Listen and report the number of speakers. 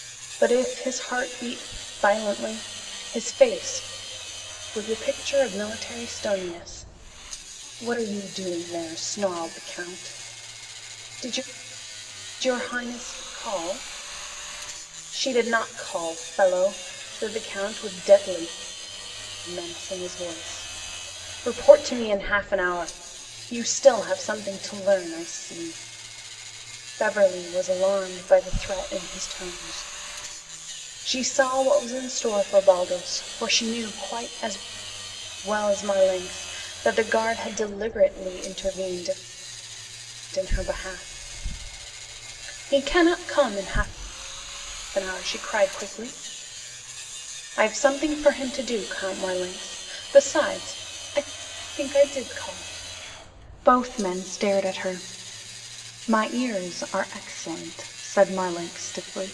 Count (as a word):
one